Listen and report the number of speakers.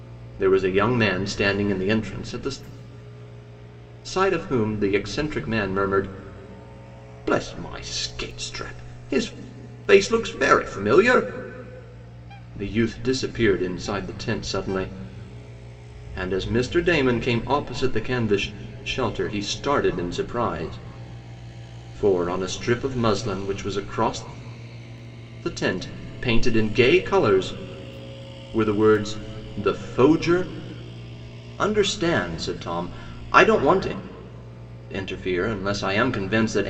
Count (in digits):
1